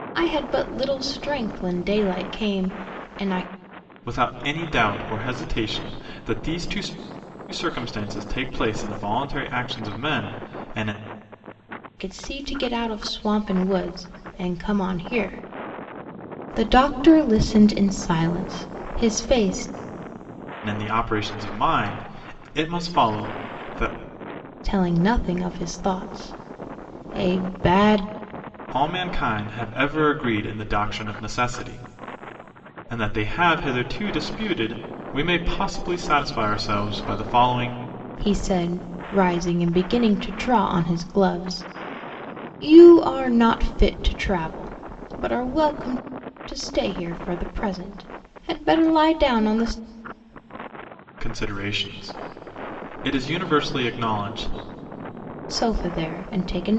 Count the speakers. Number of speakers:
2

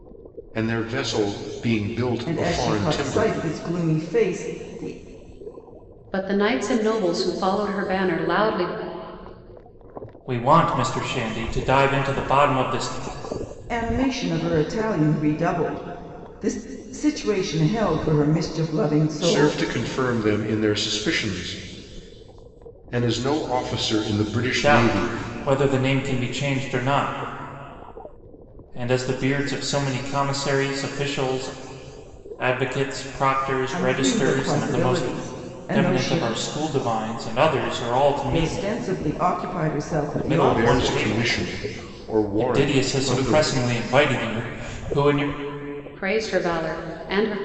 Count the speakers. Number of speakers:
4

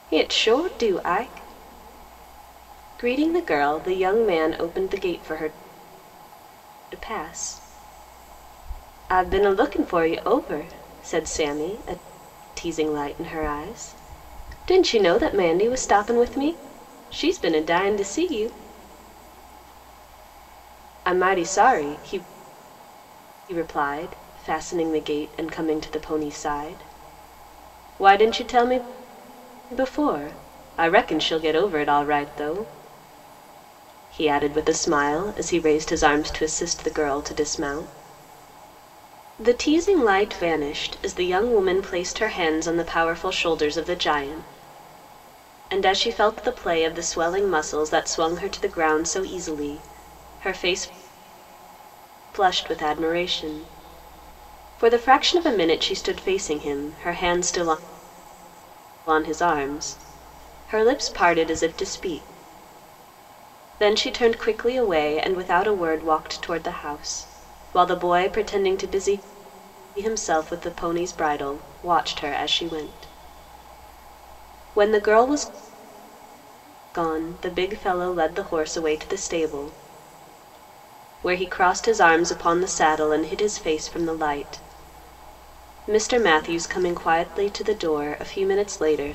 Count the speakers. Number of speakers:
1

